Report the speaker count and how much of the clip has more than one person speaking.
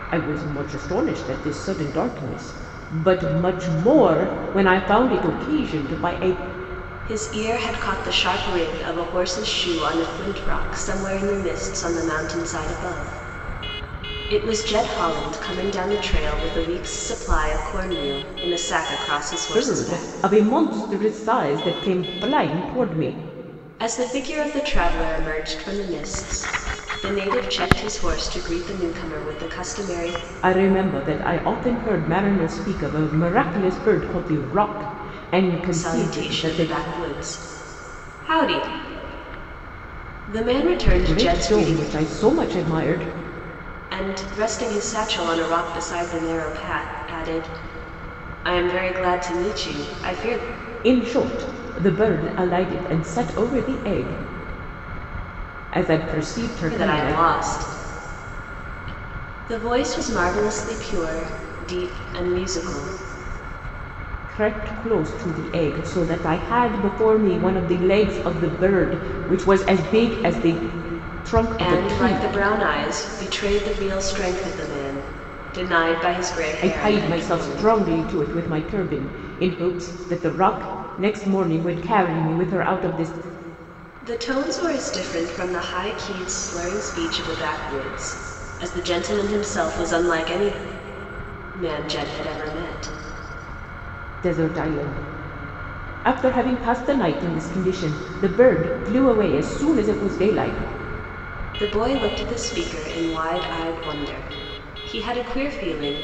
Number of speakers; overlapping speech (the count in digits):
2, about 5%